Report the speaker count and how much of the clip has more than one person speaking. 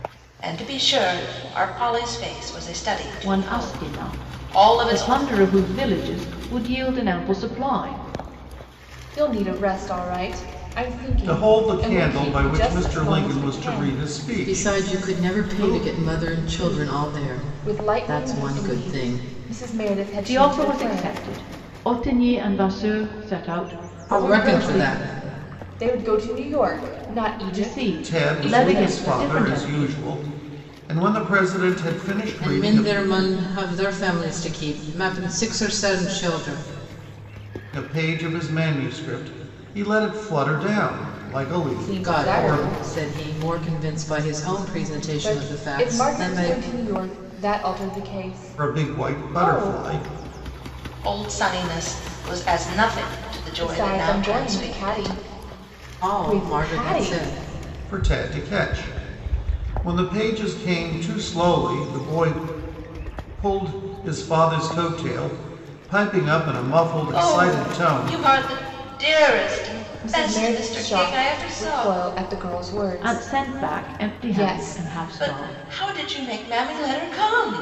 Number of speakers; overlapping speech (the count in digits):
5, about 33%